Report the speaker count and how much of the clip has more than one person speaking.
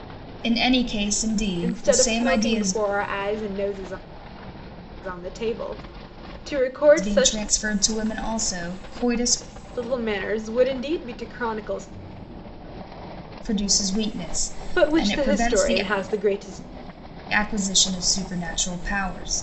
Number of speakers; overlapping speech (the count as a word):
two, about 15%